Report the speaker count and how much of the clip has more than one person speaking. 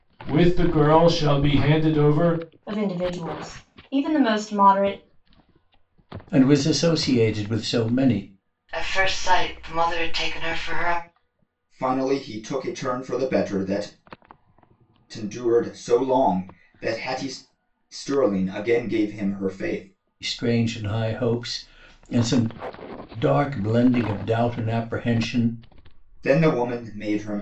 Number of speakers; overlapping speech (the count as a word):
five, no overlap